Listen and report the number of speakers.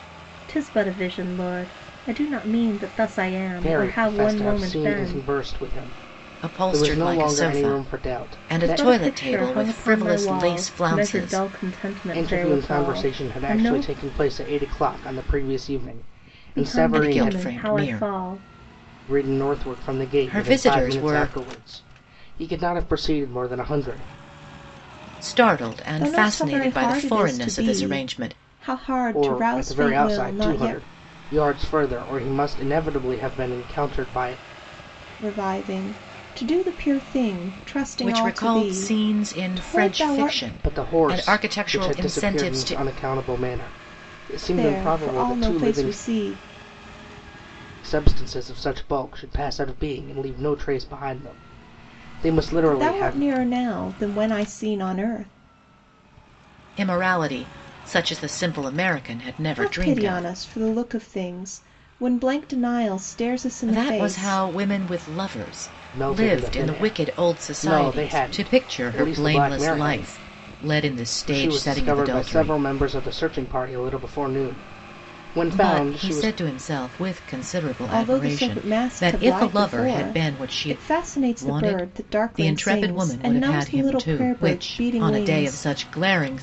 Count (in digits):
3